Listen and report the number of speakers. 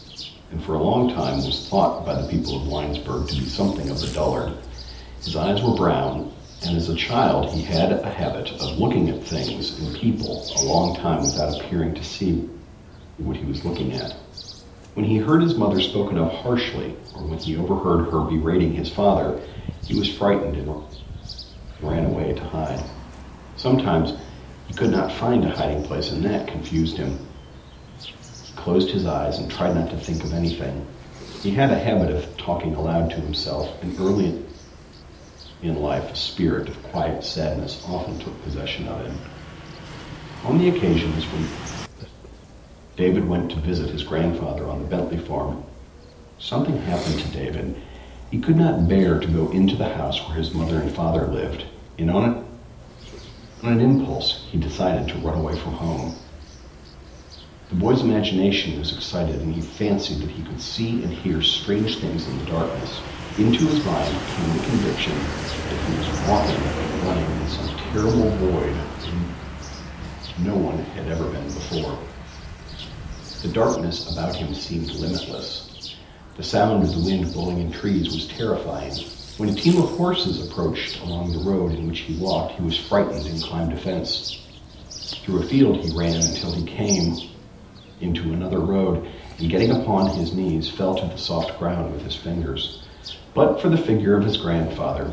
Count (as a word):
one